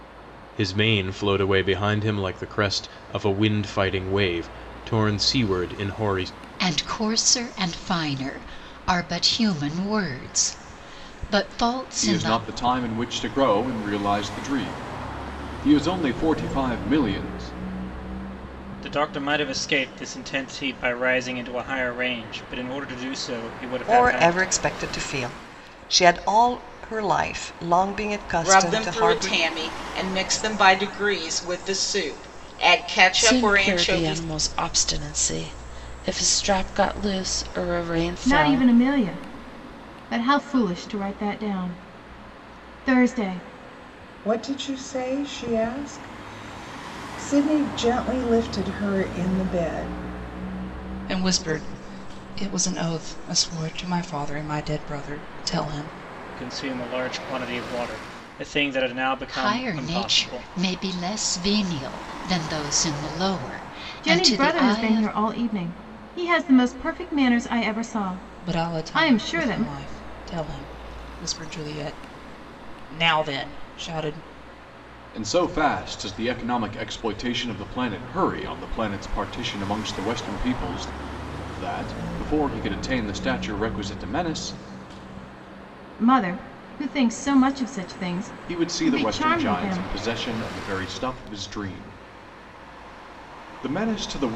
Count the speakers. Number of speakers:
ten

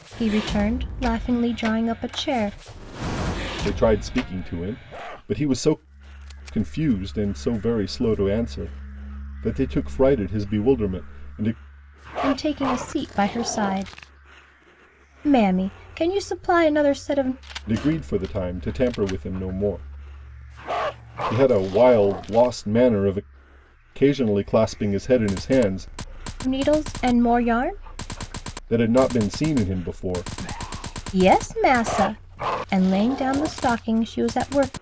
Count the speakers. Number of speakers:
two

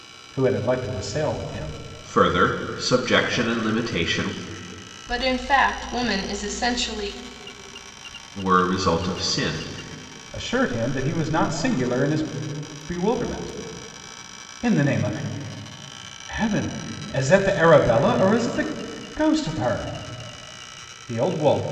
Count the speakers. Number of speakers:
three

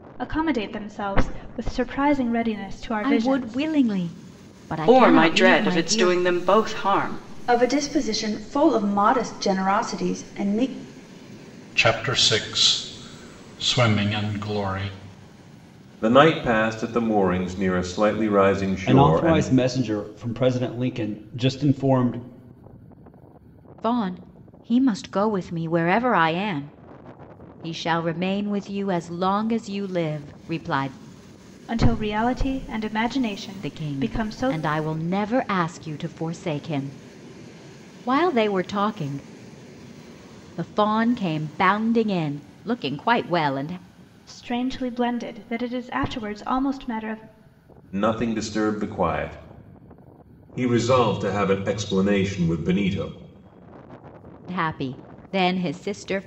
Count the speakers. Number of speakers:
seven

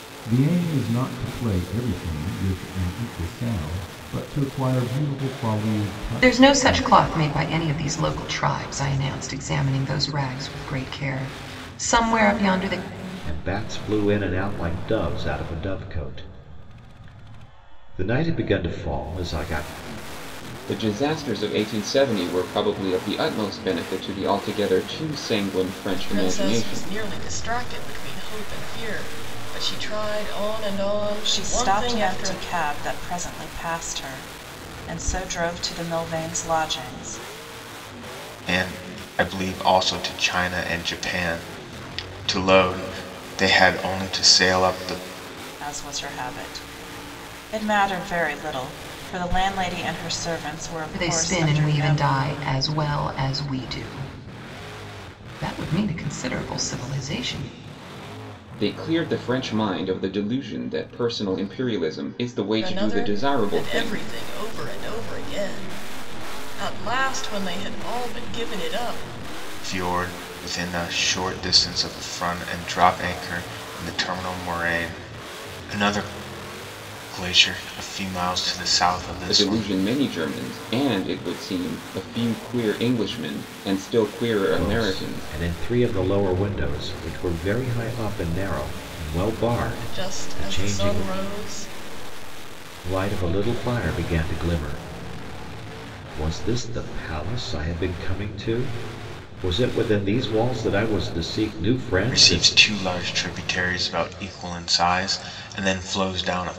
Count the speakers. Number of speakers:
seven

